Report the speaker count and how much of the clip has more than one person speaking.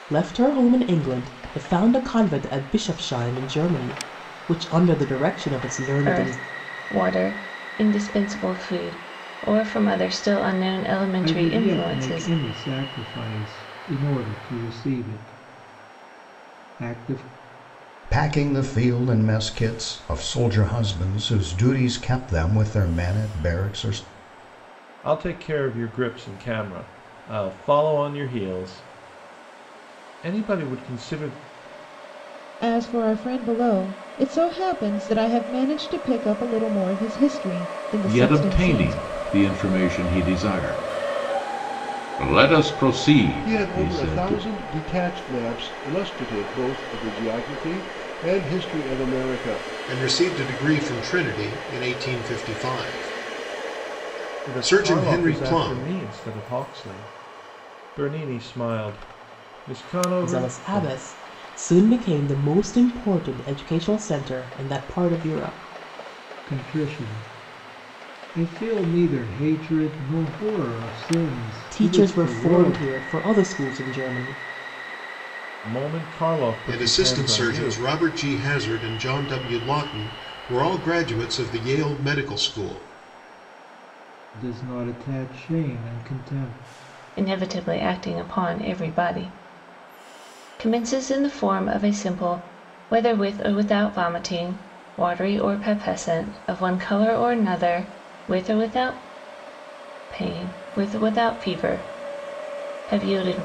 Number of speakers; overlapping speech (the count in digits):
9, about 8%